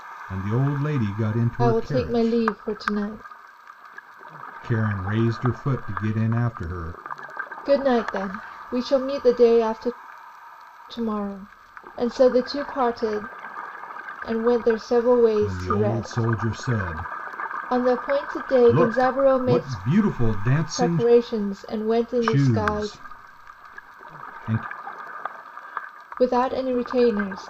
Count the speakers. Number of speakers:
2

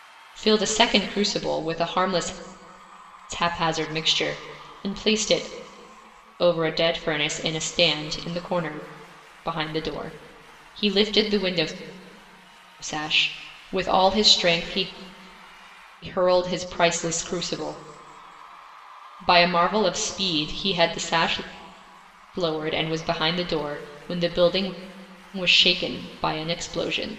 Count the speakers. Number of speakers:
1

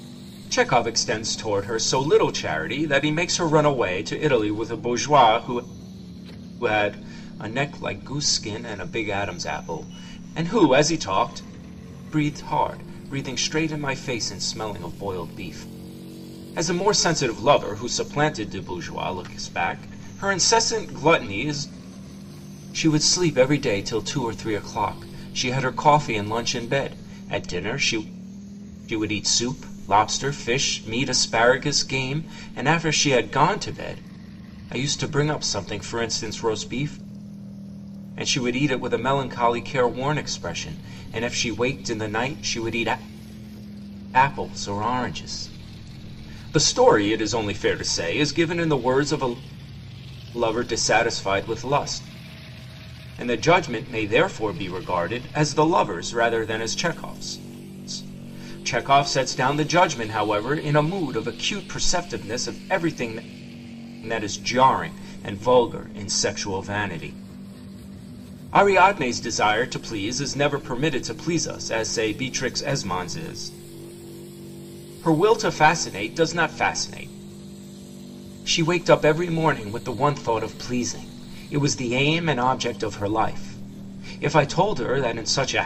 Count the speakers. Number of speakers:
1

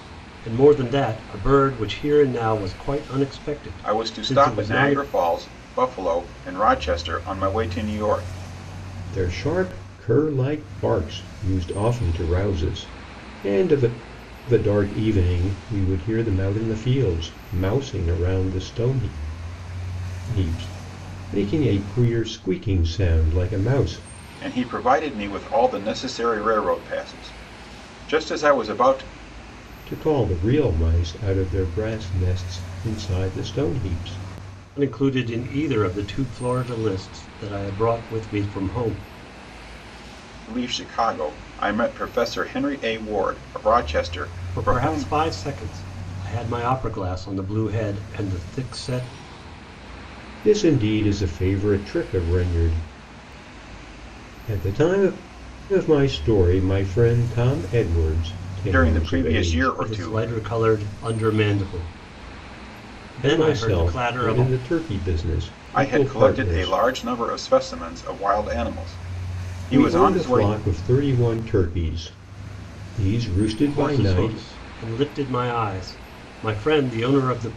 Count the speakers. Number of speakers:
3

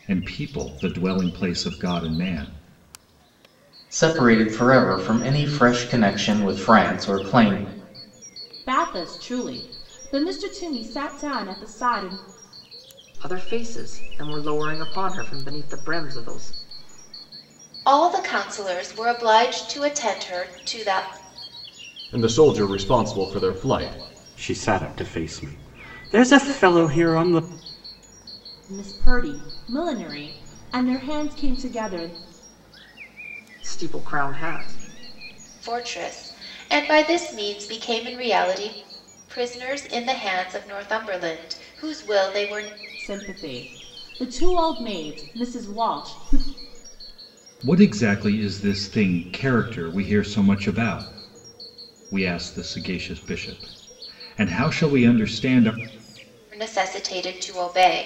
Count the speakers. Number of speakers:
7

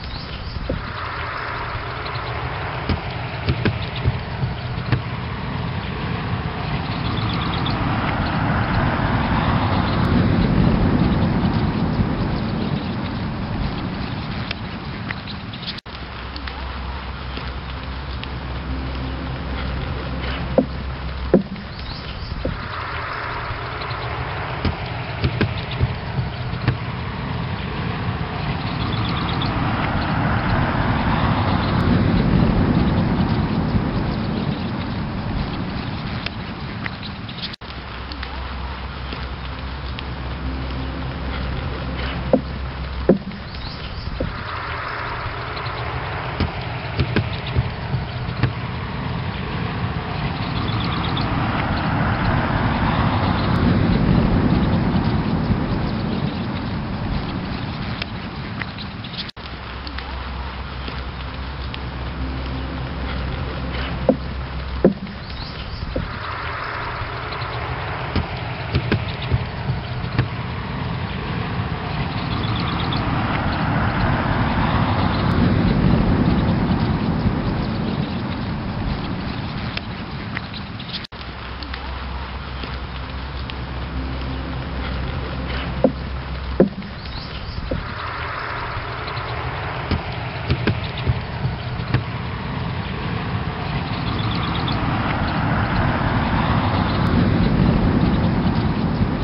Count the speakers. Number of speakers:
0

